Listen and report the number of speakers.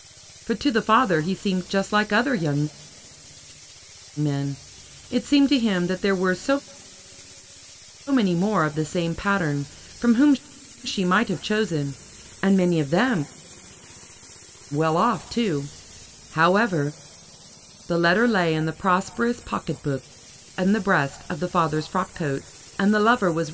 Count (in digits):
1